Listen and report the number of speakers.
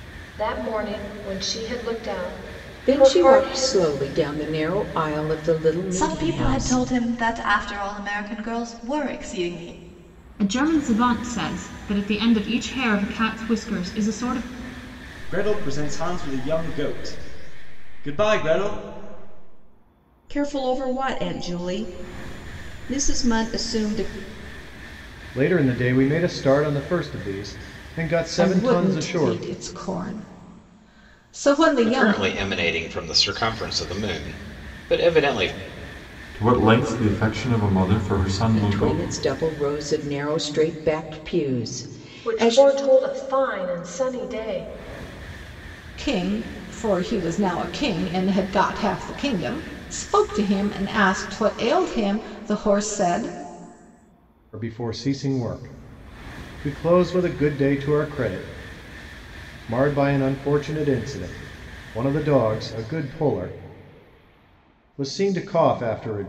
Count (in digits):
10